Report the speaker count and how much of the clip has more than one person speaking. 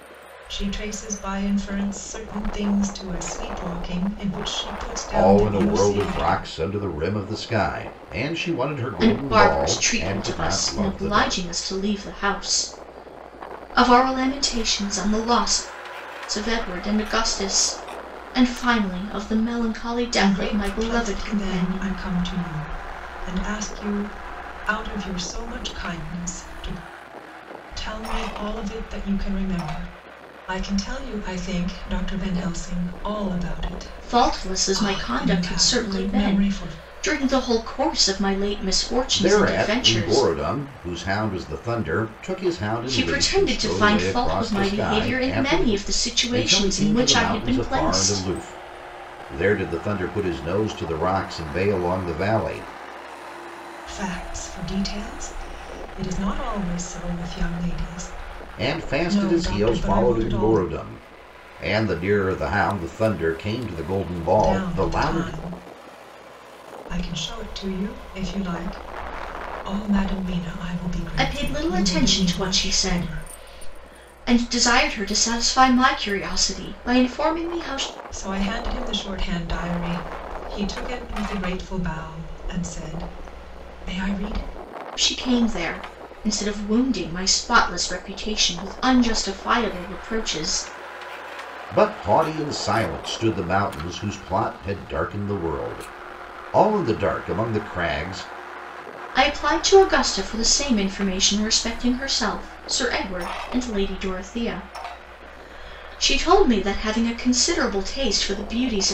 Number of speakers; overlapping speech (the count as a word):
three, about 18%